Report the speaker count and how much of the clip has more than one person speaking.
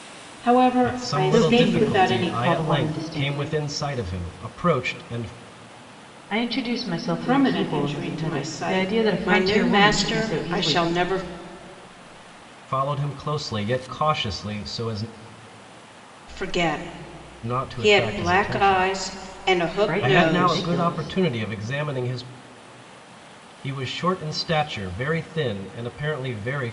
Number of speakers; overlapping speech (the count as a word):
three, about 34%